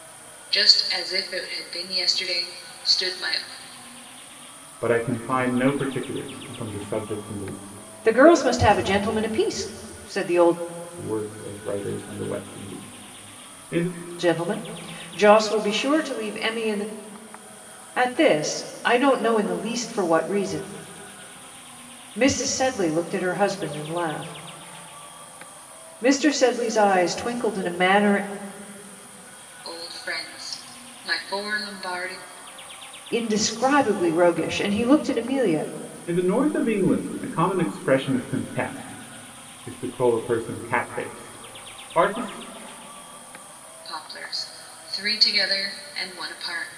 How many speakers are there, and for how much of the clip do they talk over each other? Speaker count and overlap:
3, no overlap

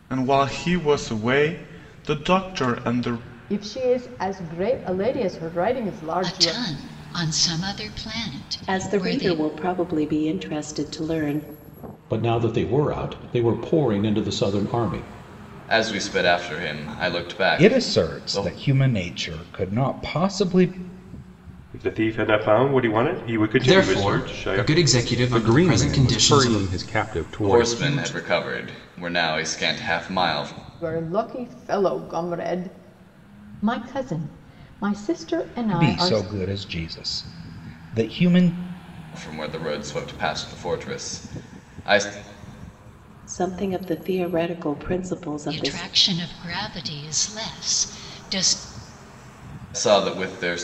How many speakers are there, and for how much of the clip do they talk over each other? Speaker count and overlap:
10, about 12%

